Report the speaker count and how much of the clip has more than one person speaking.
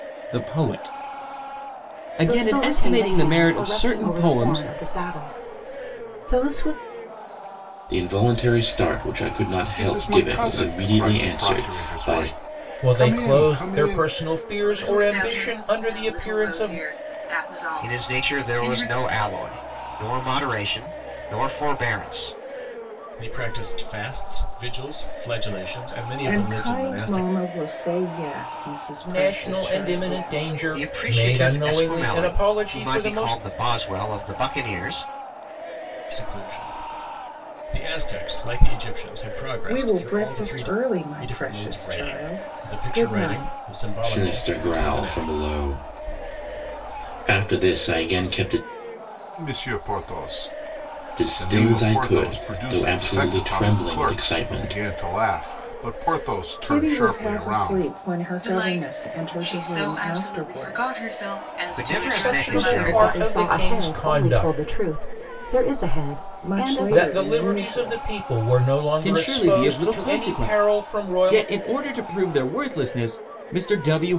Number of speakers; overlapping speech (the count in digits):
9, about 47%